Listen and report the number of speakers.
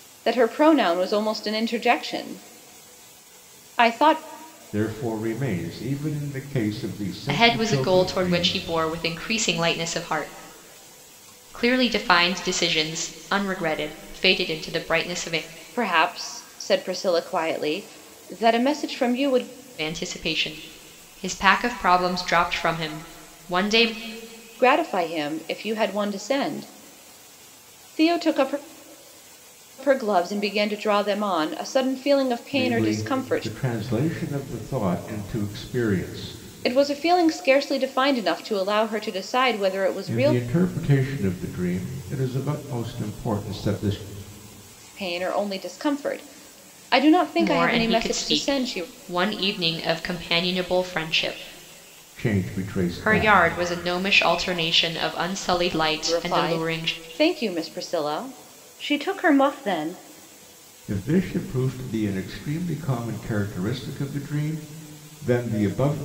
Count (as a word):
three